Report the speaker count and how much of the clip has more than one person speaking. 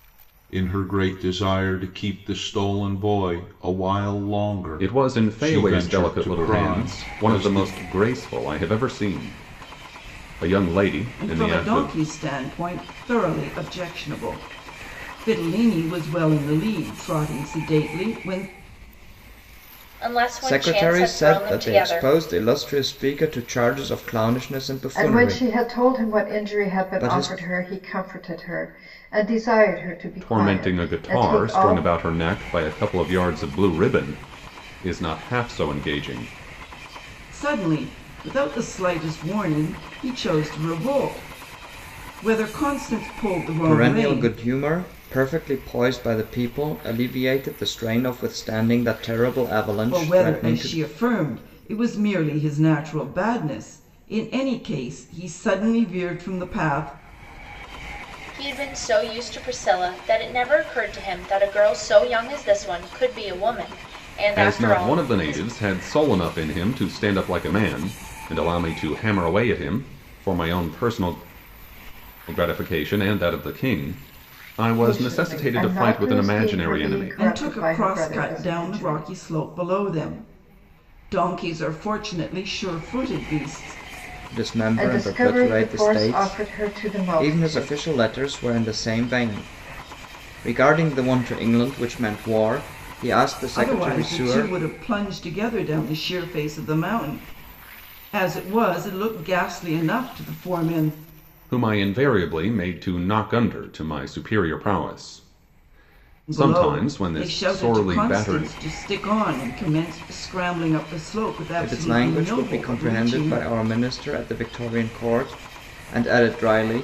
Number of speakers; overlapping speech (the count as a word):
six, about 21%